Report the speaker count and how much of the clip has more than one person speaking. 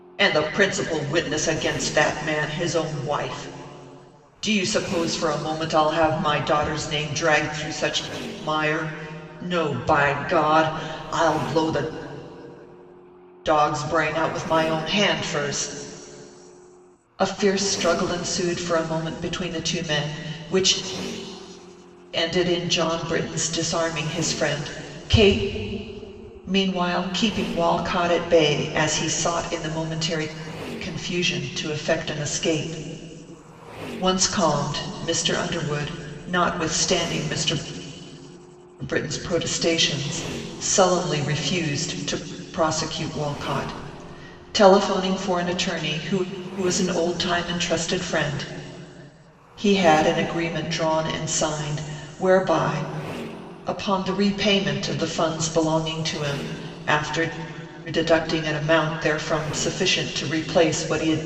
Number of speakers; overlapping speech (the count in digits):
1, no overlap